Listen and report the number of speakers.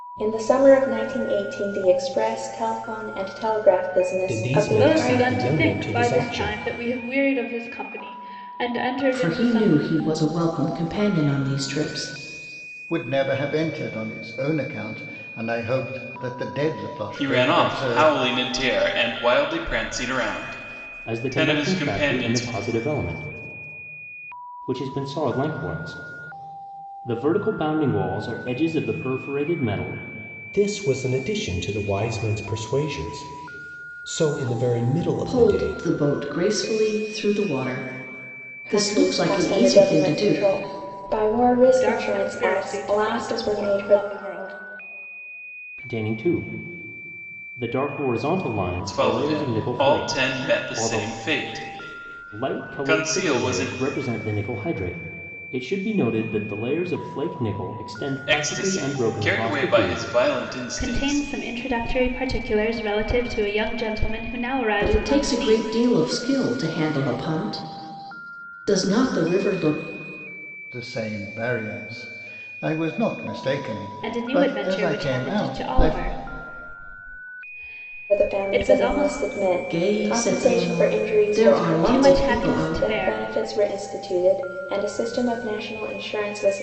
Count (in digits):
7